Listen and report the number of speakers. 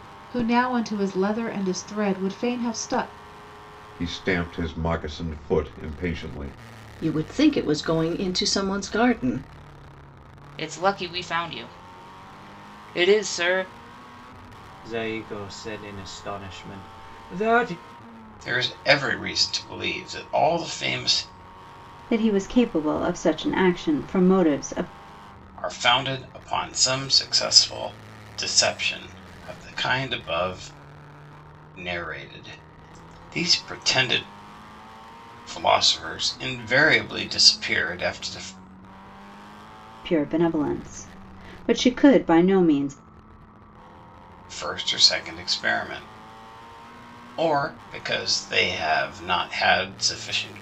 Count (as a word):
seven